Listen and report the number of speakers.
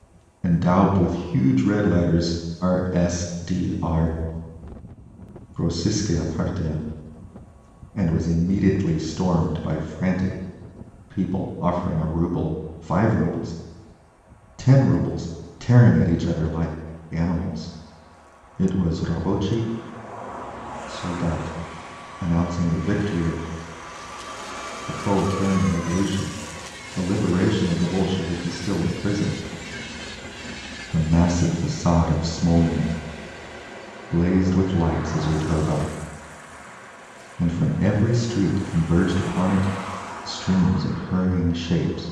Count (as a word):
one